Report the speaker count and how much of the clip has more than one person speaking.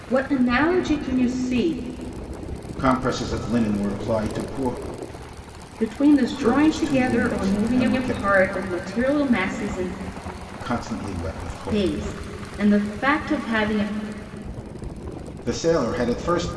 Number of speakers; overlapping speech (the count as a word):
two, about 17%